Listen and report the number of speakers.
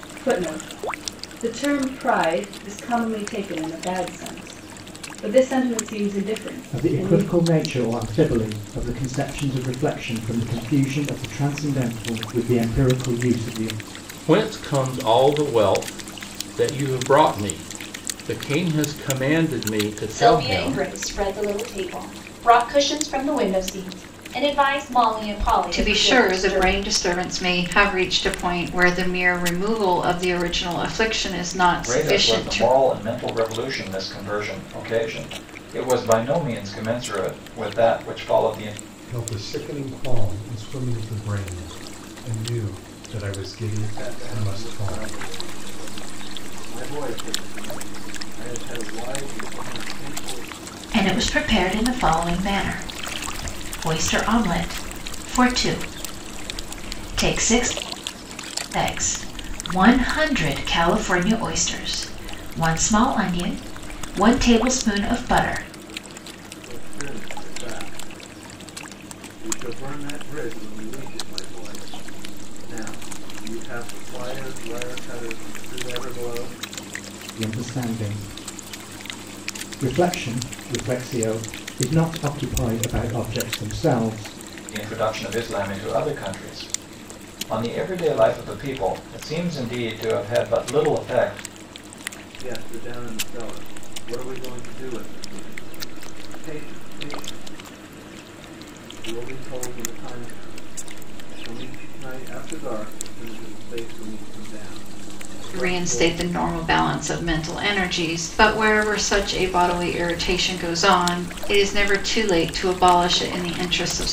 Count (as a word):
nine